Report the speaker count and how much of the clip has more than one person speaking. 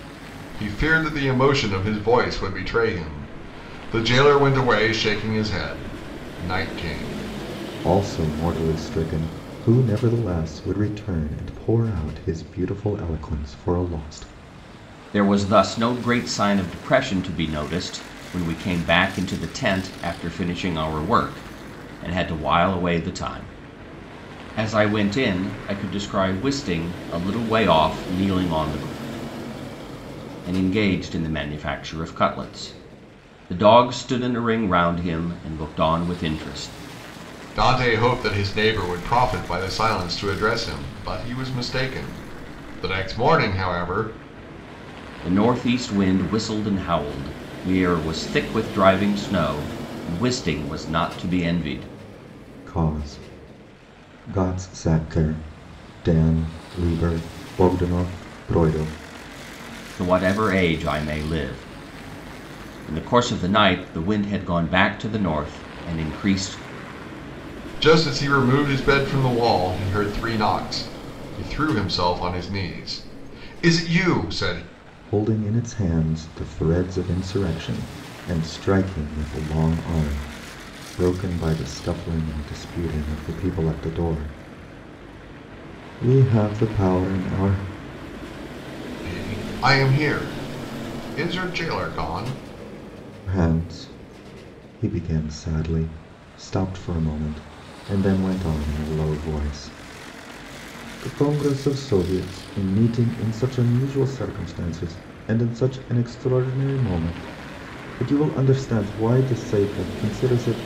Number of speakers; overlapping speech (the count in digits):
3, no overlap